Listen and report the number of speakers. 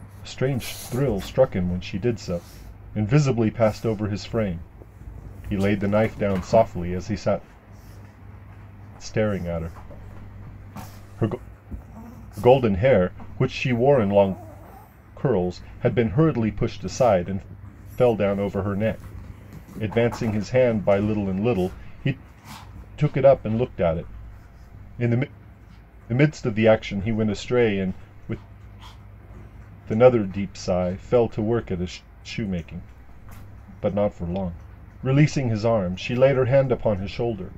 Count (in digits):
1